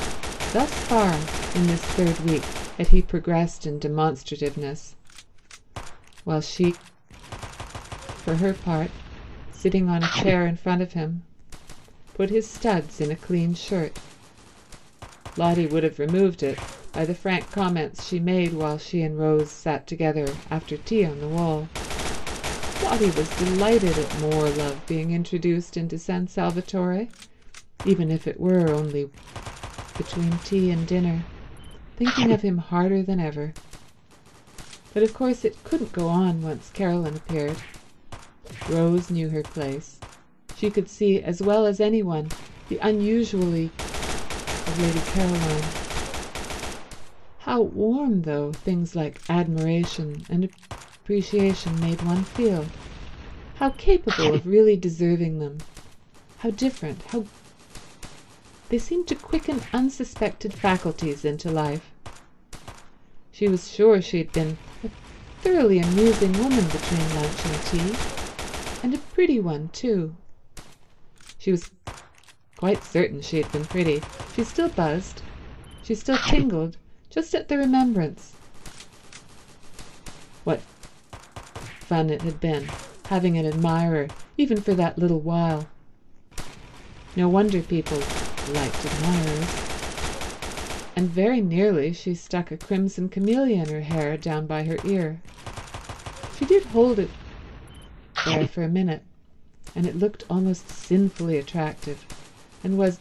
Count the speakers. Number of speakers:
1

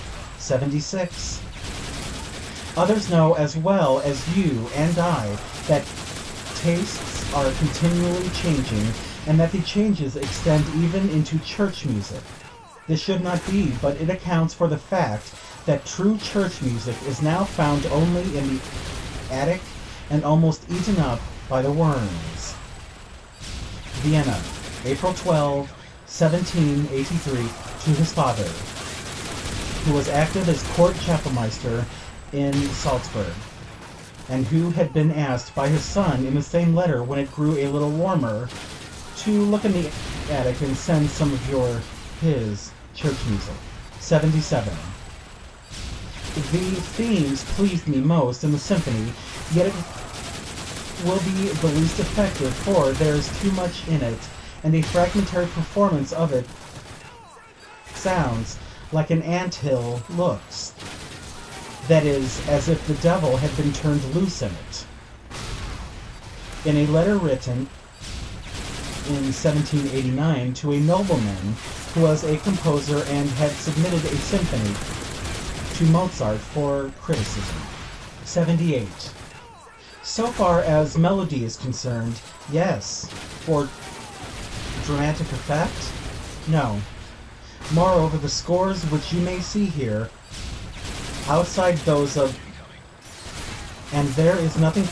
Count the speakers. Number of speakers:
1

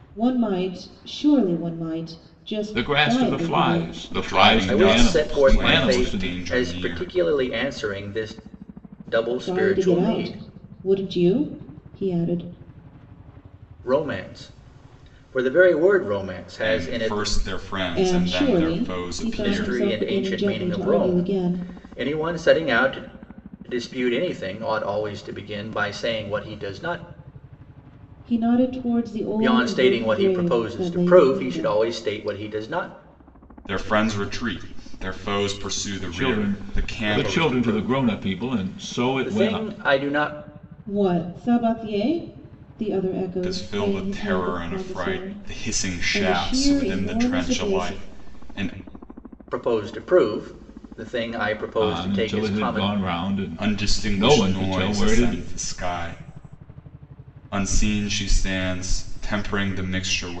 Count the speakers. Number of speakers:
4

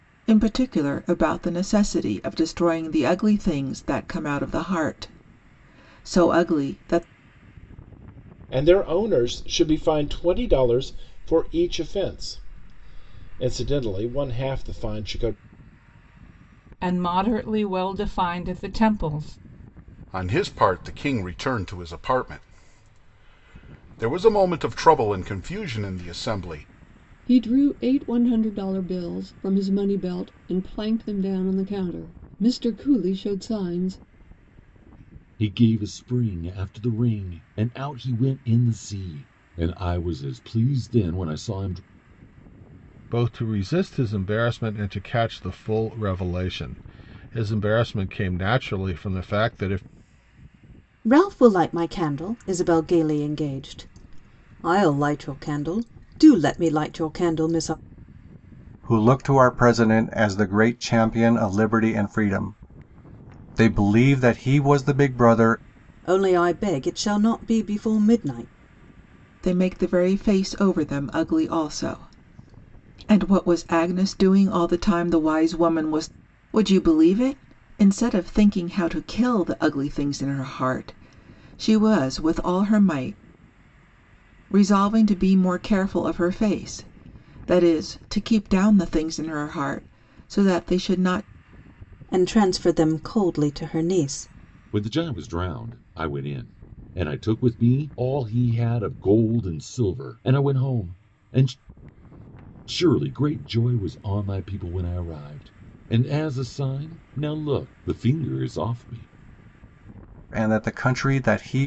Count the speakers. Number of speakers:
9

